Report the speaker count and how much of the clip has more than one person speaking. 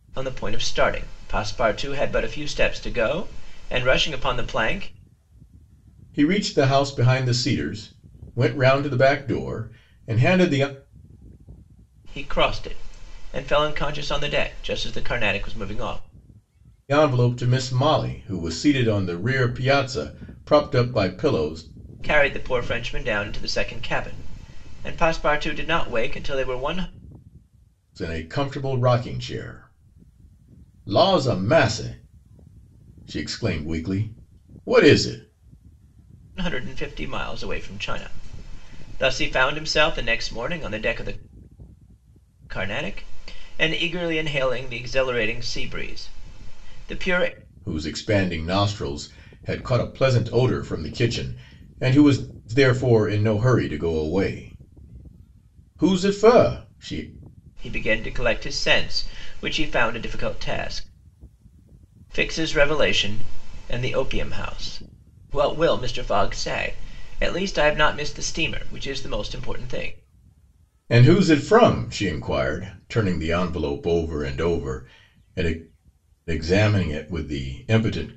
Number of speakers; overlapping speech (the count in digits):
2, no overlap